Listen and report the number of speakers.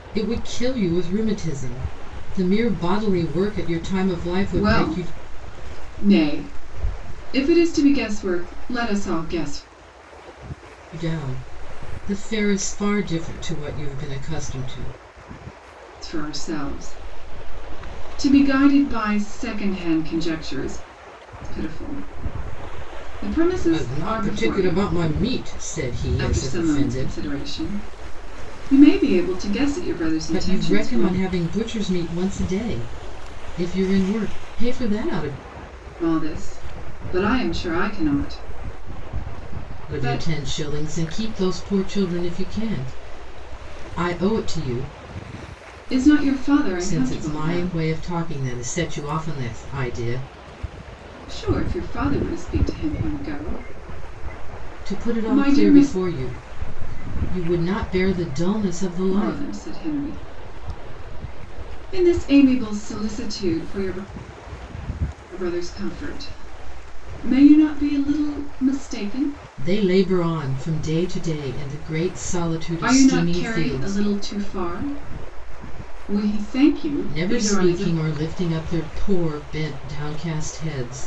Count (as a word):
two